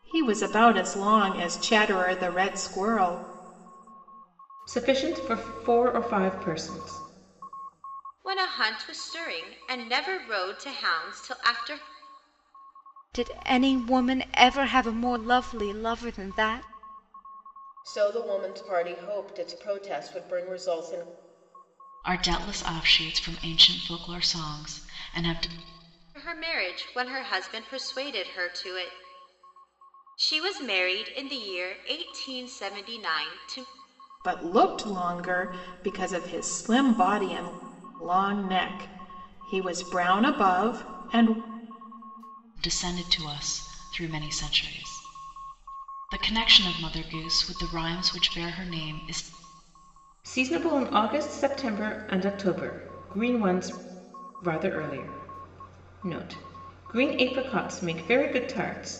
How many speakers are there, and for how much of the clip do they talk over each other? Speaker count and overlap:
6, no overlap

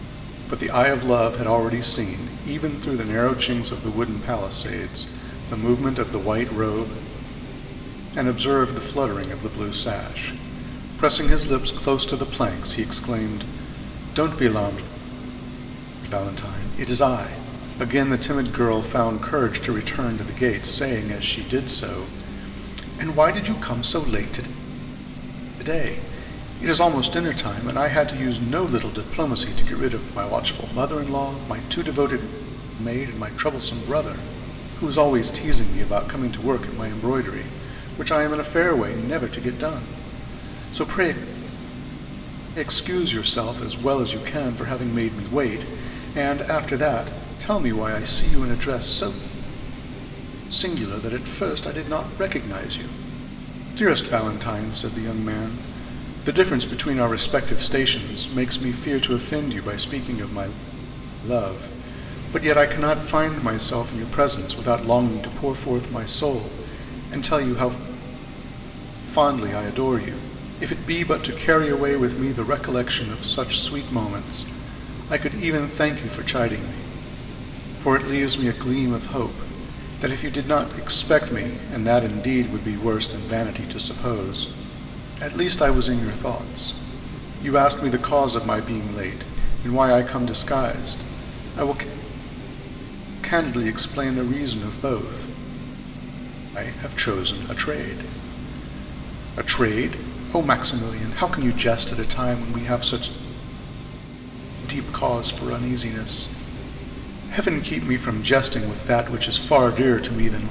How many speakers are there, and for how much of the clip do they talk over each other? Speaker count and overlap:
1, no overlap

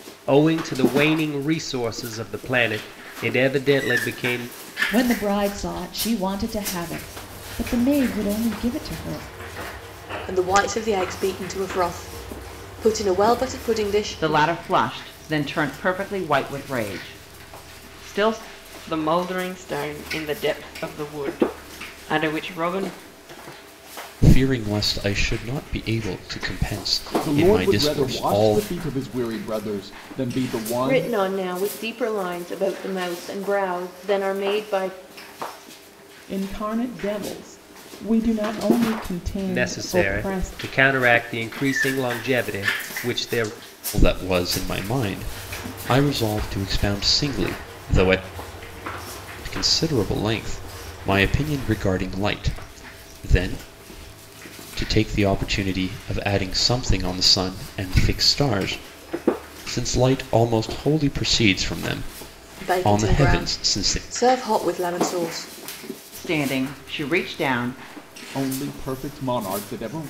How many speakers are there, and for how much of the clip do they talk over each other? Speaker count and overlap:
9, about 7%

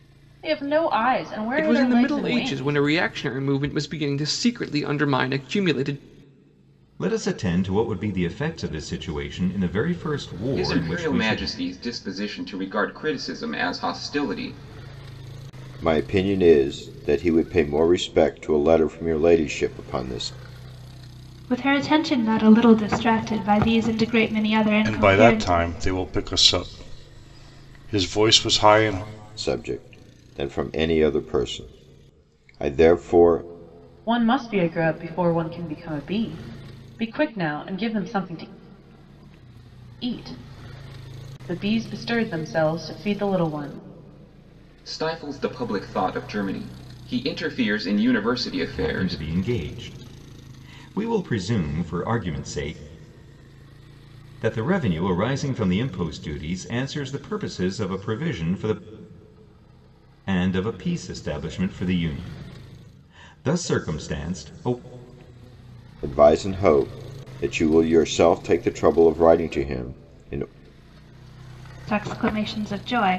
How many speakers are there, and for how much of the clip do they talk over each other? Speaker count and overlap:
7, about 5%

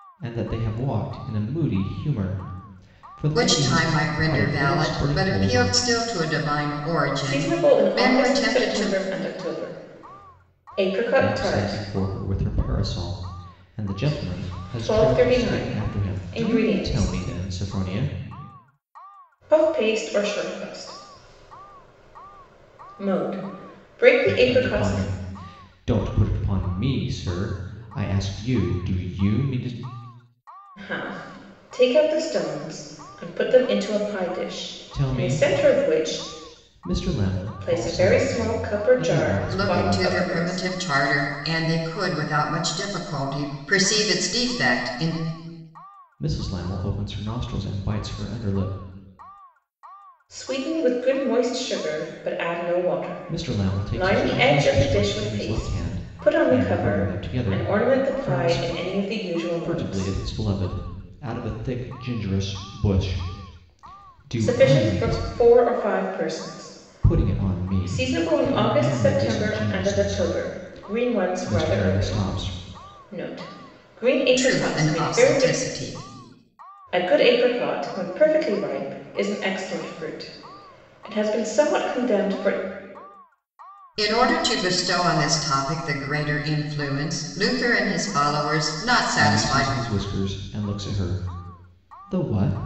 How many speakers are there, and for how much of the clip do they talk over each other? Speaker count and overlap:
3, about 30%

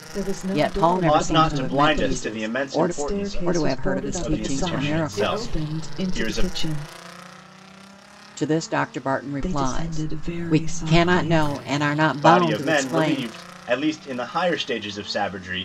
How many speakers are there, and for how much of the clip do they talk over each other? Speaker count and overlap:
3, about 58%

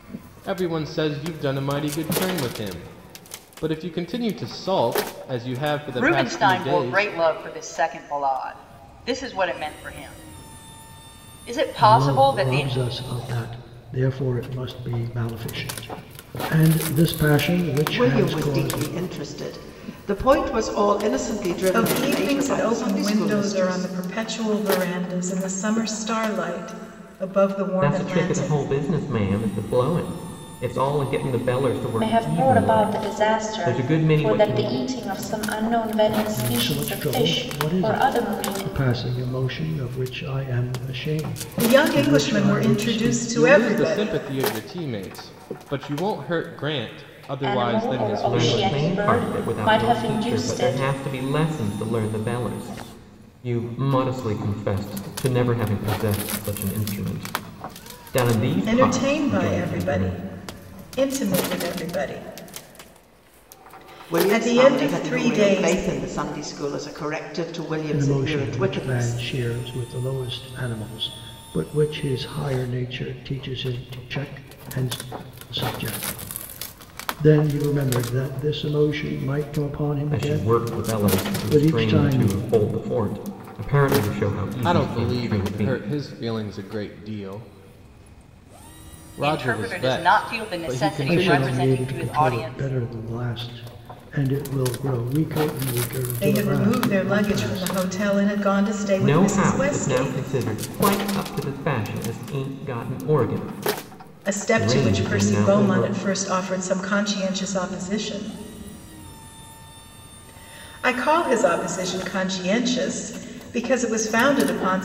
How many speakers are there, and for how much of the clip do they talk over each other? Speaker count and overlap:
7, about 29%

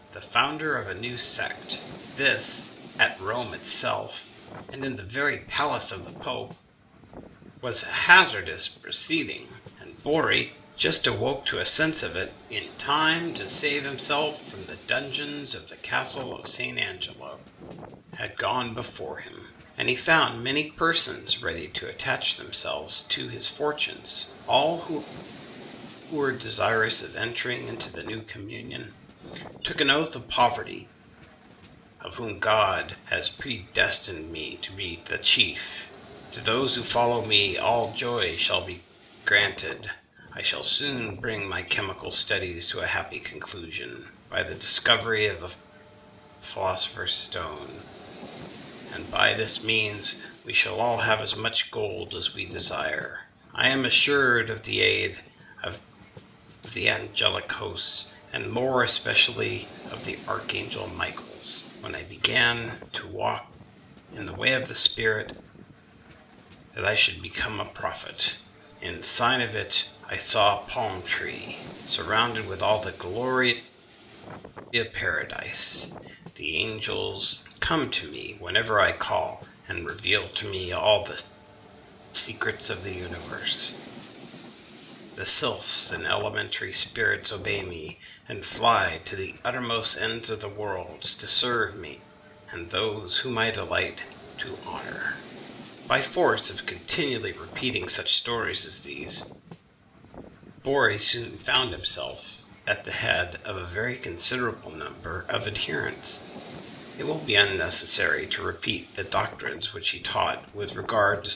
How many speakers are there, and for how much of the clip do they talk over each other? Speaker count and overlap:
1, no overlap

